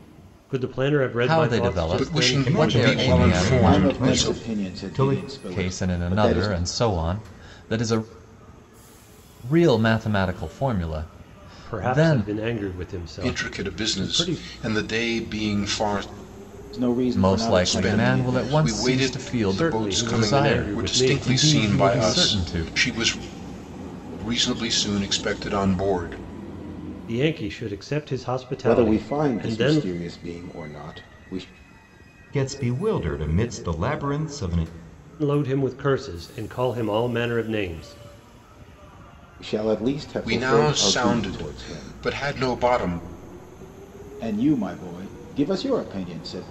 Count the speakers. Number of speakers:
five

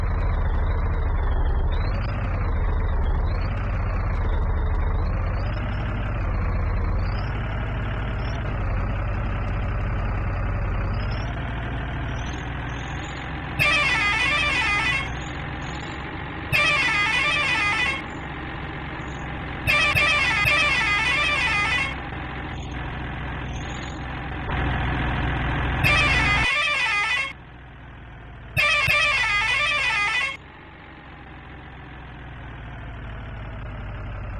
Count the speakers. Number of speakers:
zero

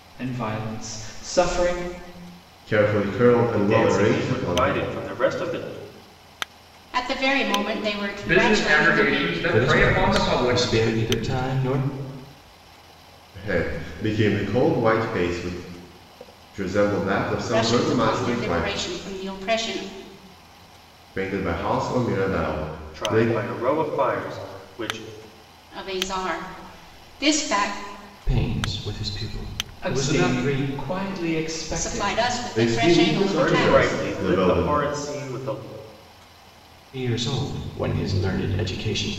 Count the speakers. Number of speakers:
six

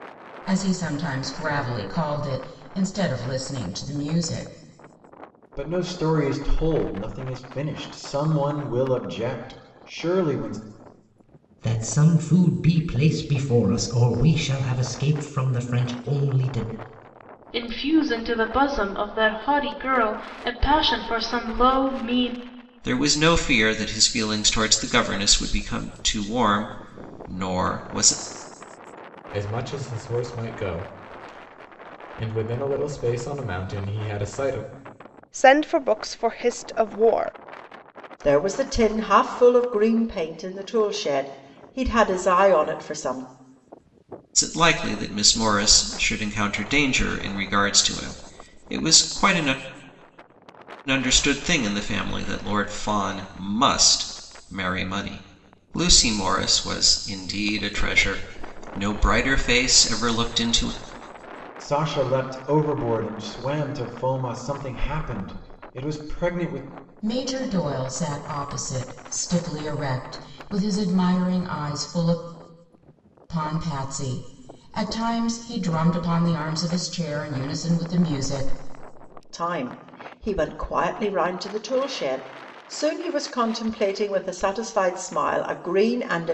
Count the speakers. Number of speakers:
eight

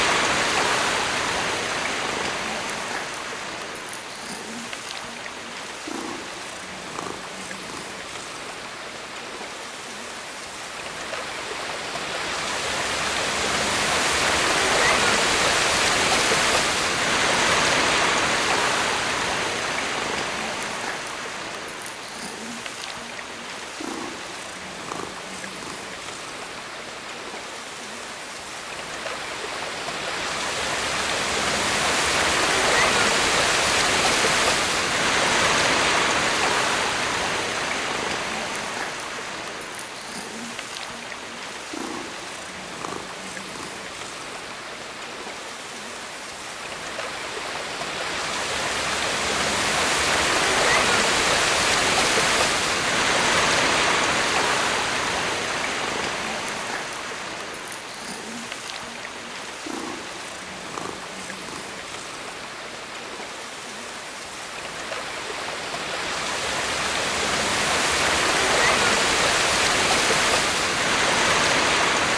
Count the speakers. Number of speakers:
zero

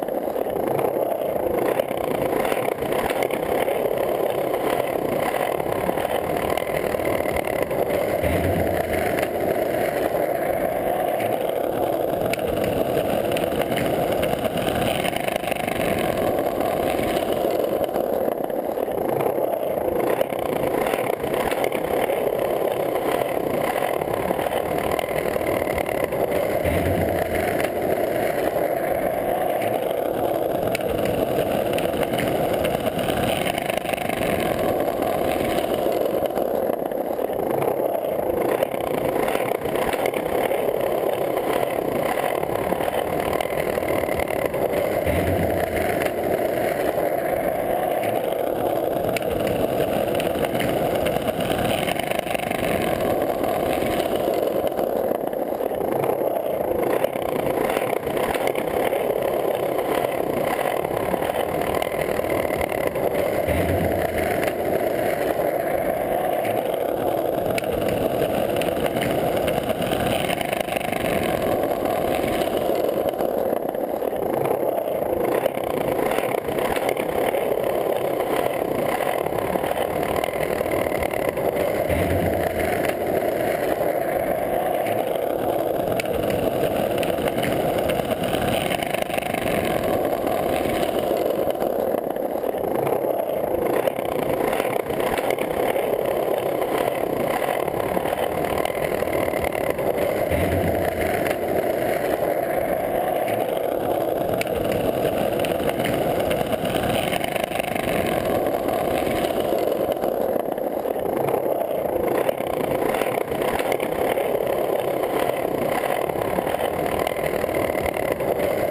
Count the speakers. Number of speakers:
zero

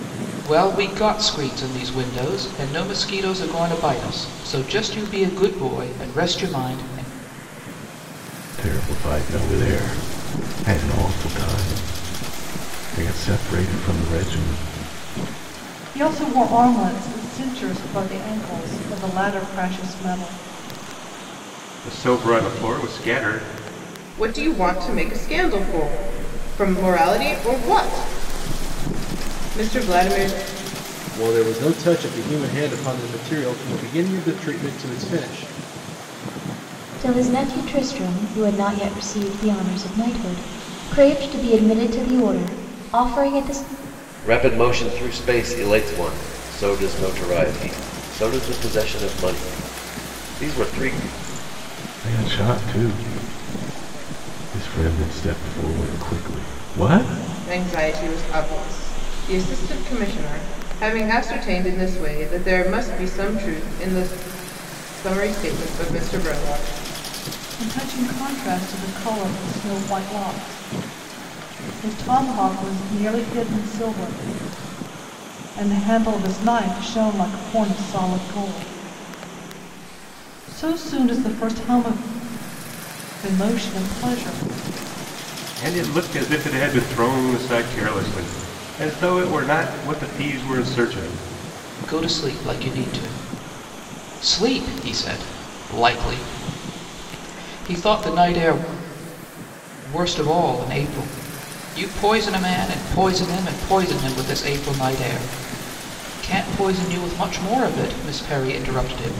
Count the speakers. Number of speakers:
eight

